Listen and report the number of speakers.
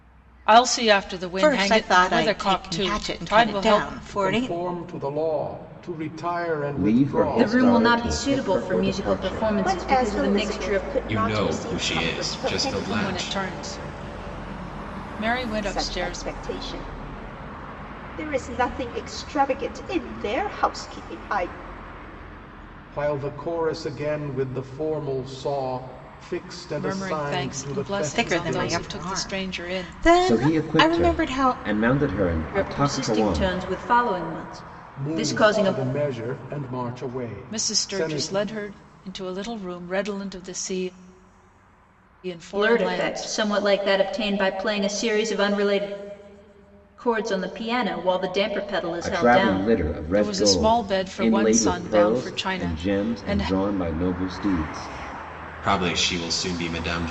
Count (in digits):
7